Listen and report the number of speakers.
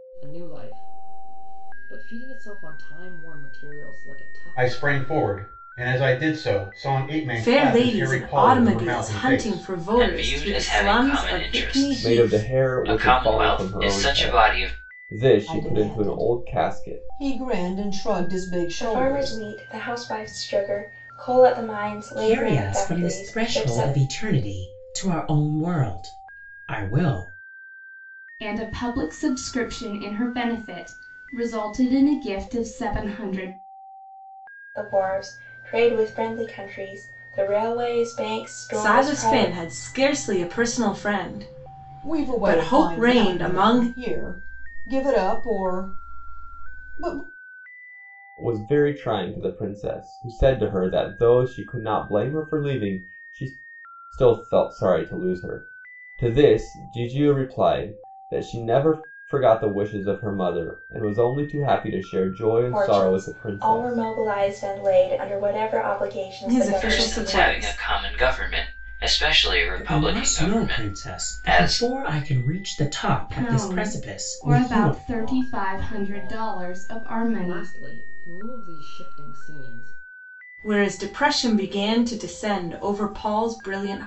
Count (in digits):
9